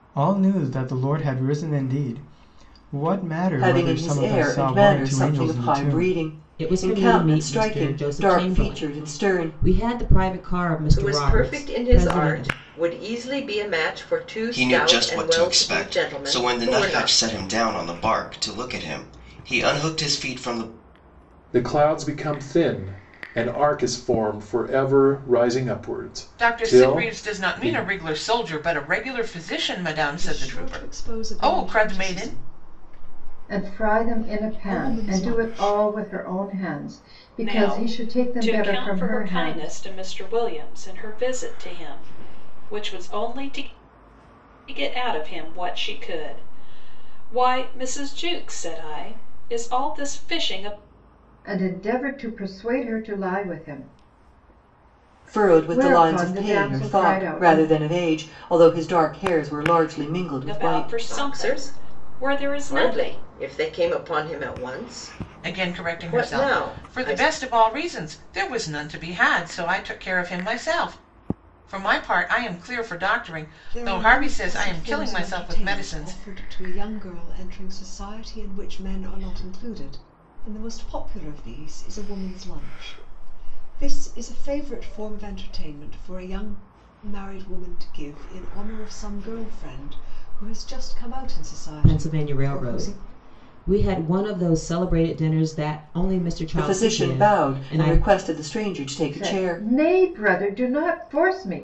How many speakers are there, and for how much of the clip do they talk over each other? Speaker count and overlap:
10, about 31%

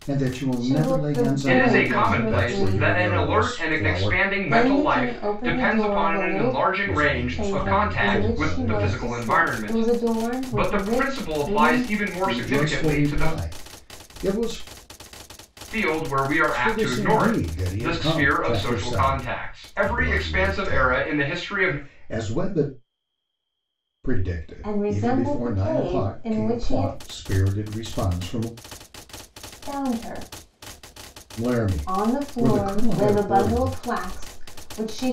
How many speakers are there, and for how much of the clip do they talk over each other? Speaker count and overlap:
3, about 62%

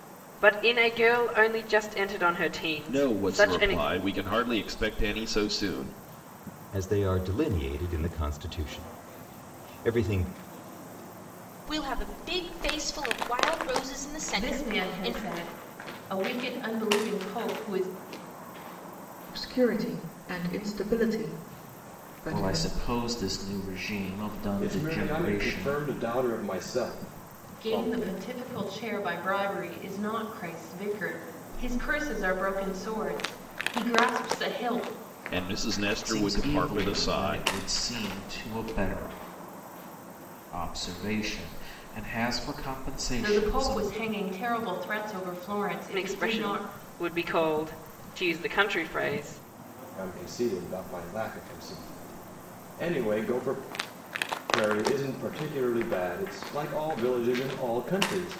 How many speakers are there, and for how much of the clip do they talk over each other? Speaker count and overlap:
8, about 12%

